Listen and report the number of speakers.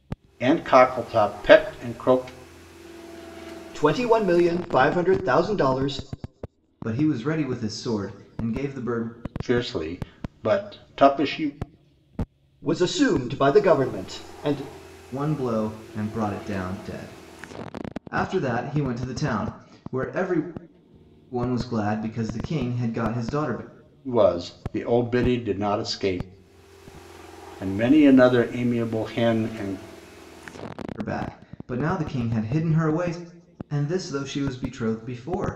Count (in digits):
3